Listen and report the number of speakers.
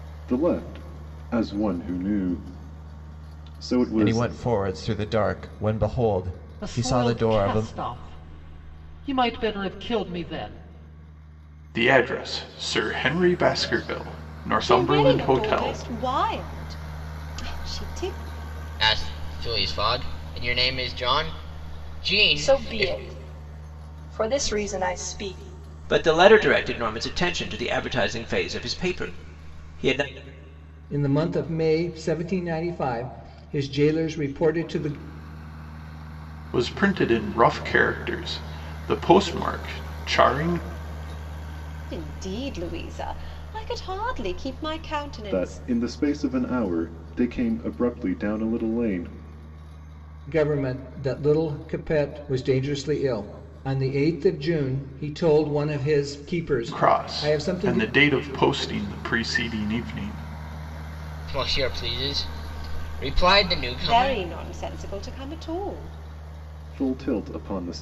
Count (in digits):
9